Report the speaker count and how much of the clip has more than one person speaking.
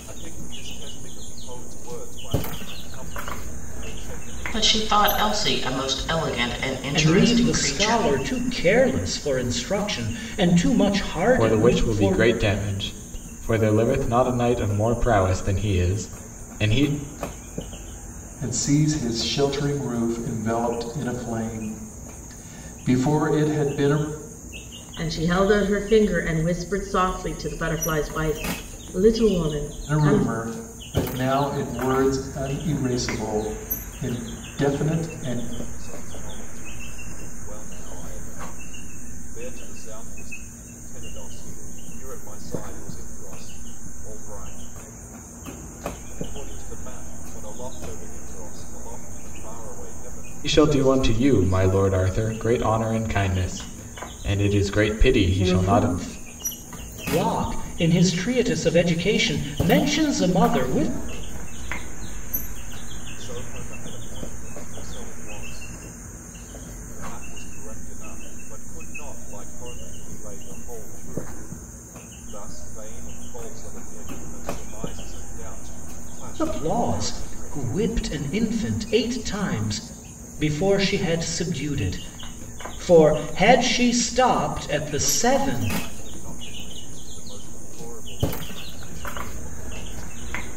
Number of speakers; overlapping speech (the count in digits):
6, about 10%